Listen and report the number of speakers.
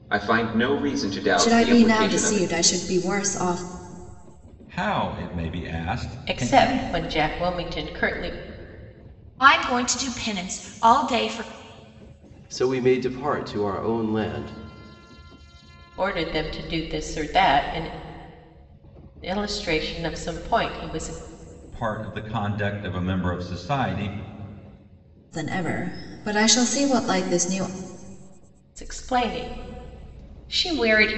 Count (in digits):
6